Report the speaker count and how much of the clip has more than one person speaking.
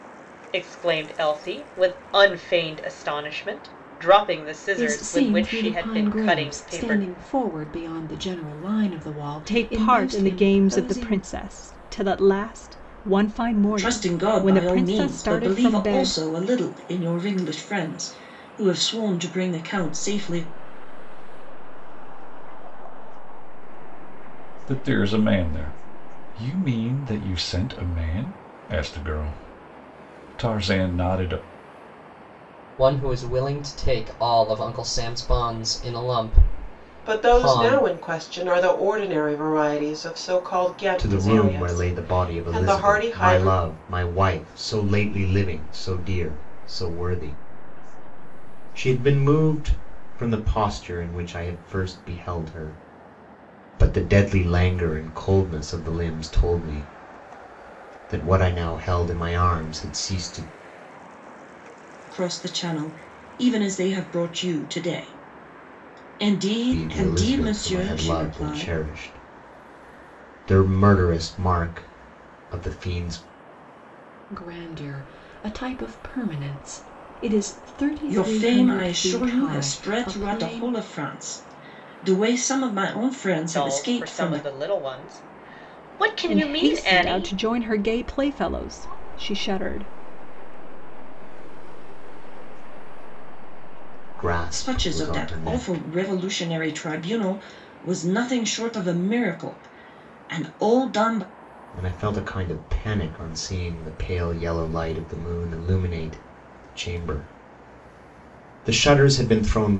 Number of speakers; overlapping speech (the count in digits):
9, about 24%